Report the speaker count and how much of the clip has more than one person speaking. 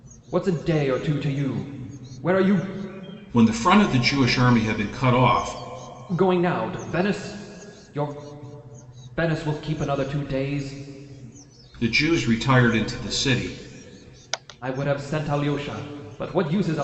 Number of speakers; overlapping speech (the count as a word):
two, no overlap